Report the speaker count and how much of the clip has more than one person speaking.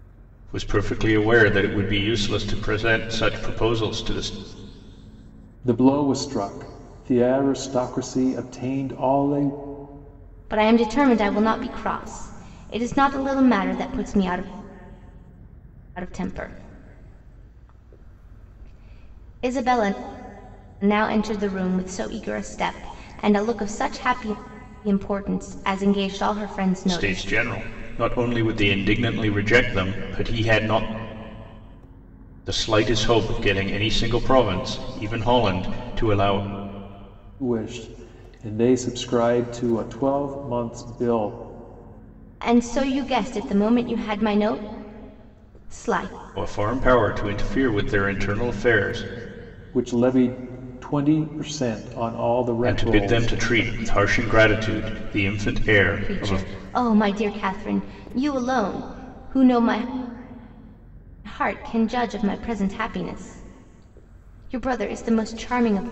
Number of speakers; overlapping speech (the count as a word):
three, about 3%